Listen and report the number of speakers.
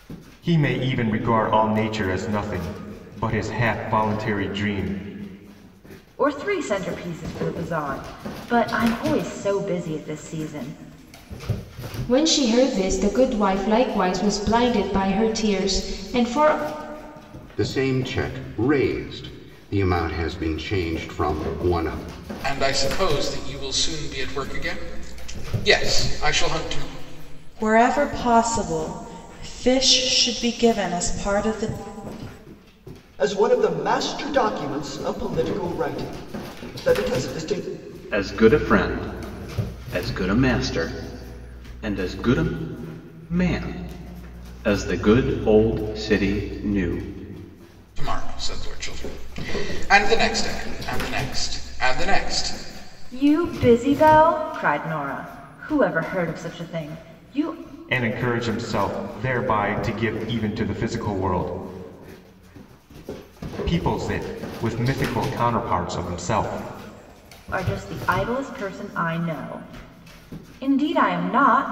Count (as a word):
eight